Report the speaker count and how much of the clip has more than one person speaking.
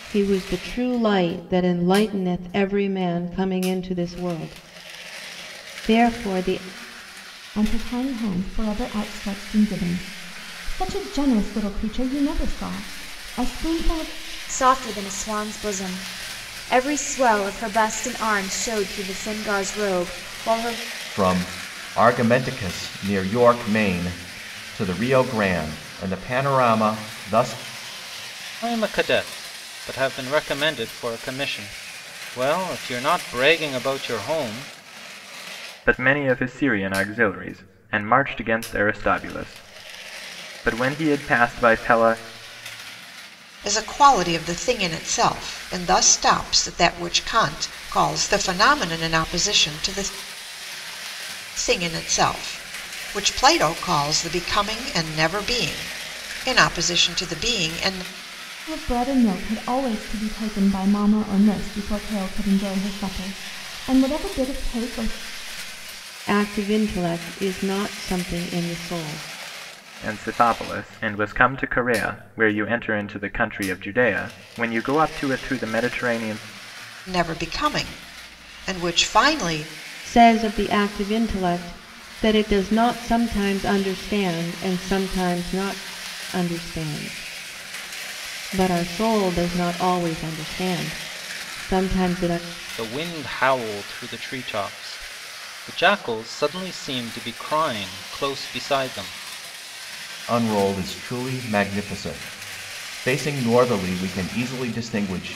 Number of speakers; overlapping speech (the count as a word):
seven, no overlap